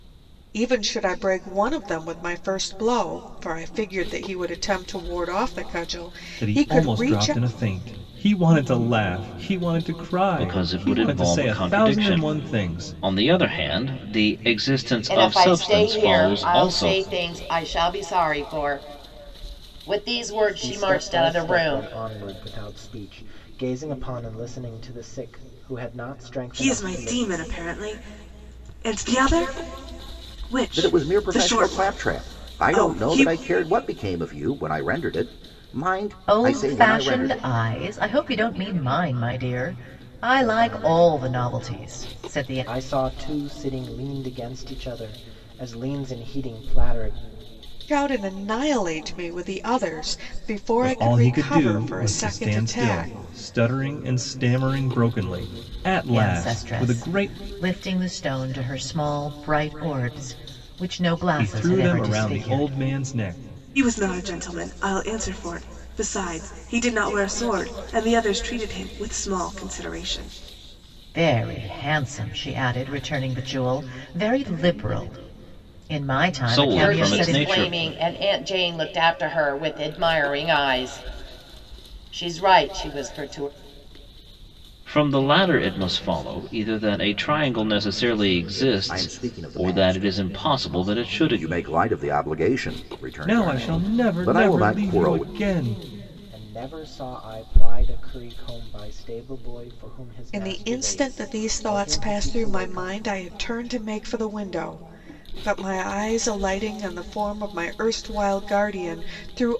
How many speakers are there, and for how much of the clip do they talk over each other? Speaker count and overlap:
8, about 26%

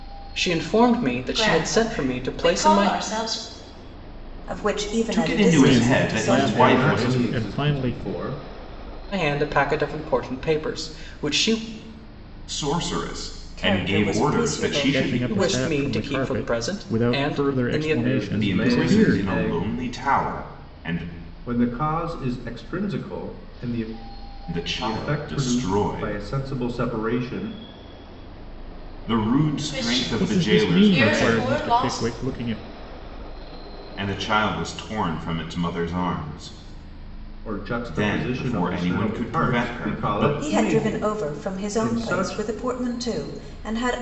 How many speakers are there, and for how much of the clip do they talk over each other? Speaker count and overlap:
6, about 44%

